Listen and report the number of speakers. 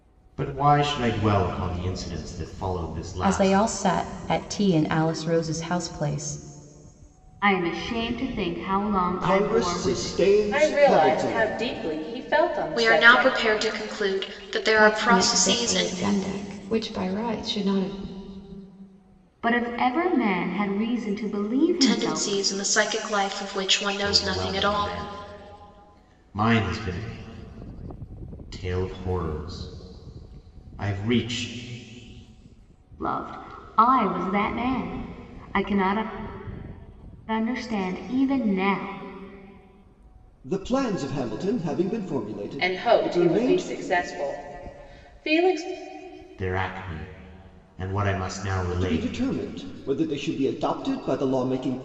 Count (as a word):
seven